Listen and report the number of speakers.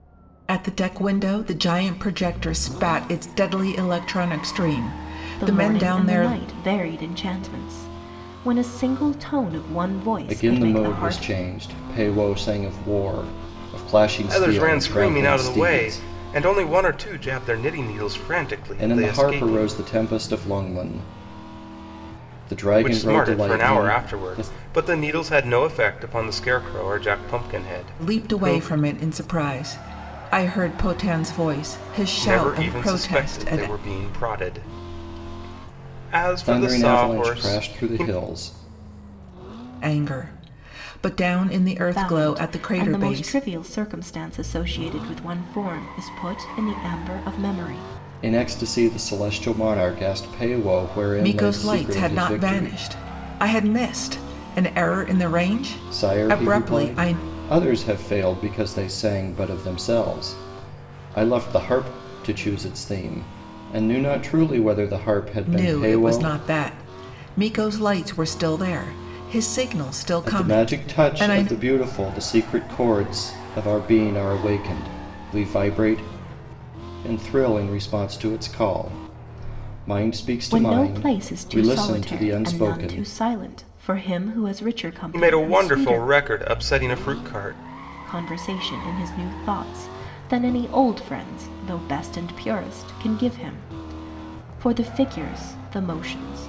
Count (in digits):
4